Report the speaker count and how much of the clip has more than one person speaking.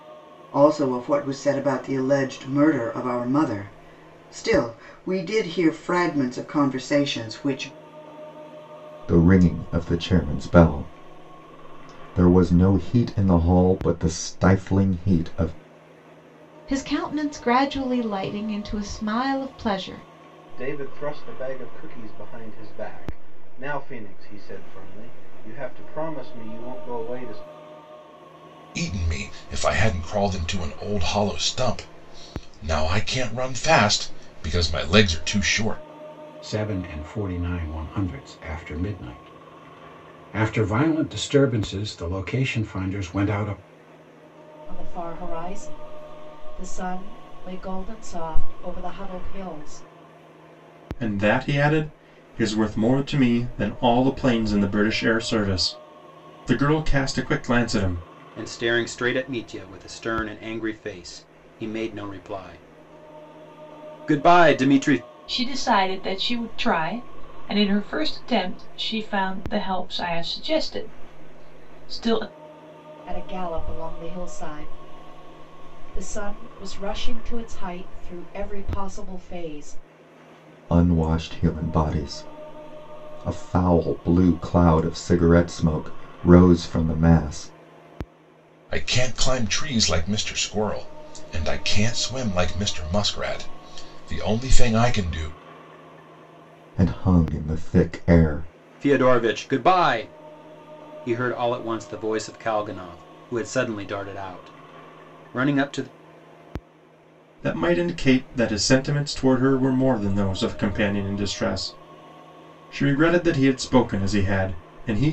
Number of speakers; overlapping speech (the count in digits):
10, no overlap